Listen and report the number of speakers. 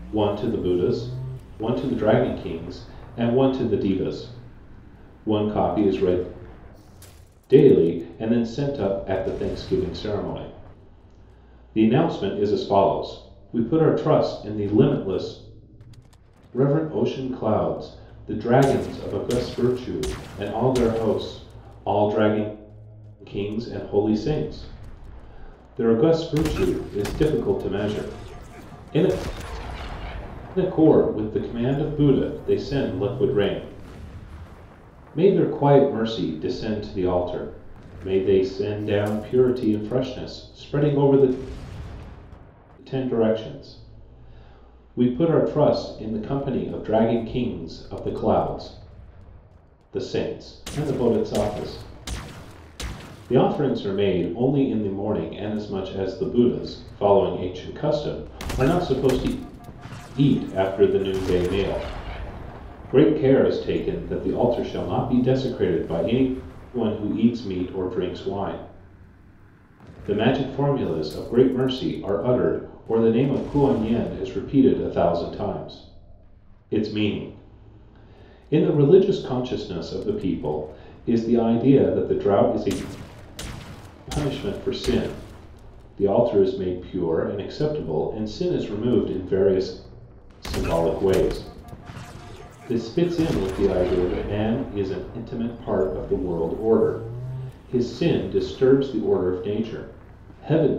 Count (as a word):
one